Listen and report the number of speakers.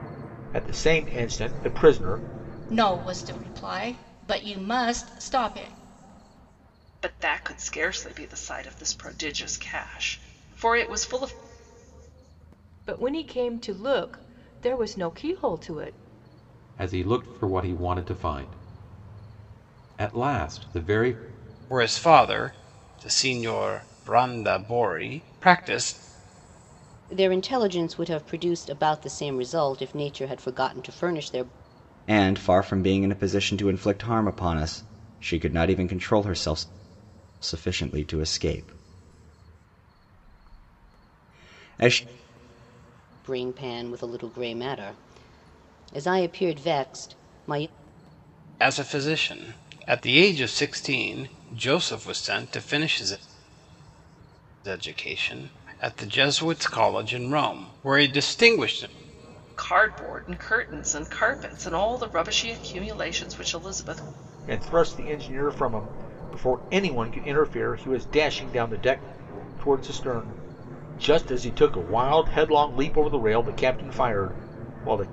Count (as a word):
eight